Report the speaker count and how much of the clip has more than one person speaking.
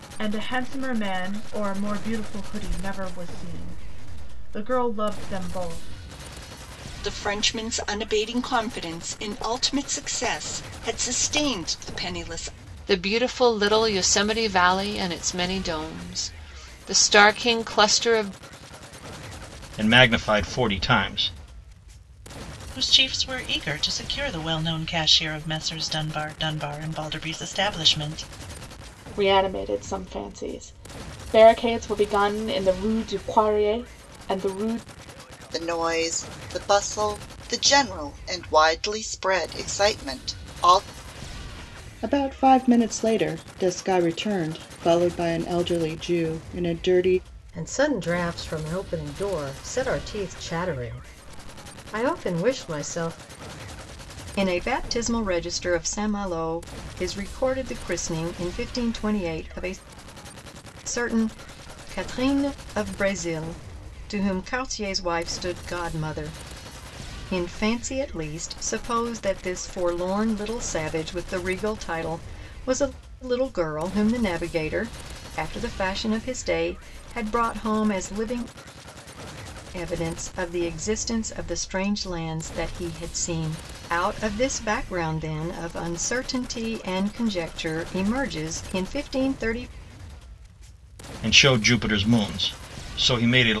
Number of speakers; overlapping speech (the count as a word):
ten, no overlap